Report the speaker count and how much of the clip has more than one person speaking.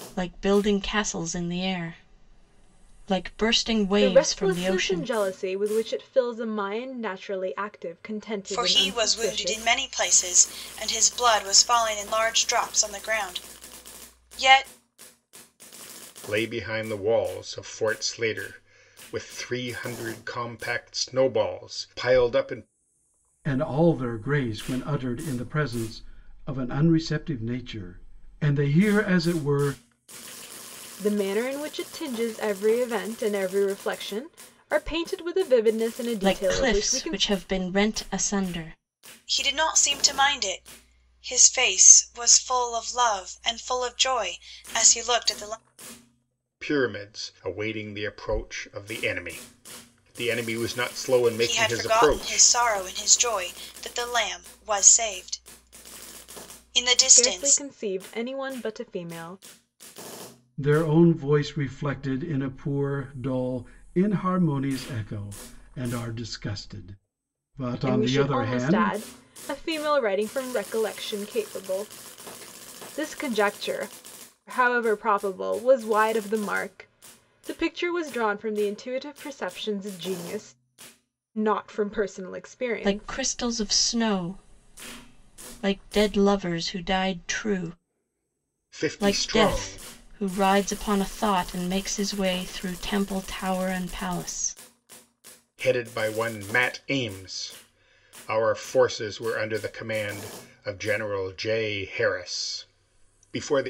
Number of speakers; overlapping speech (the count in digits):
5, about 7%